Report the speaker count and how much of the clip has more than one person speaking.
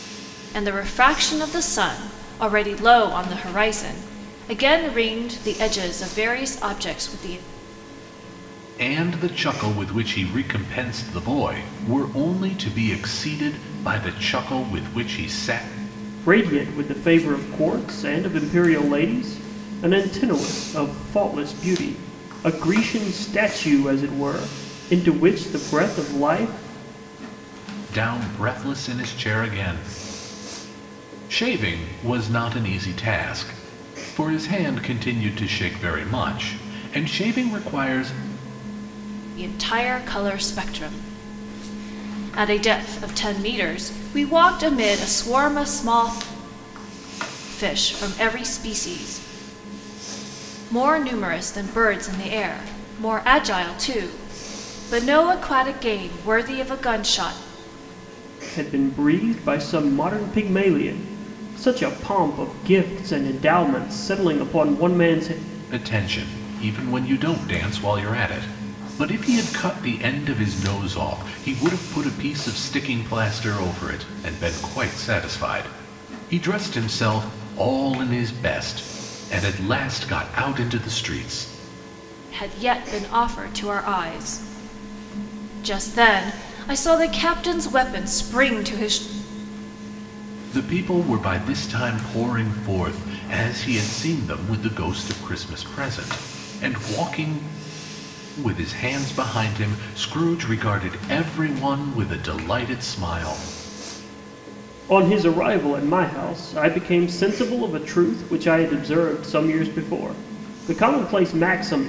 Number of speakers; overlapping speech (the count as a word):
three, no overlap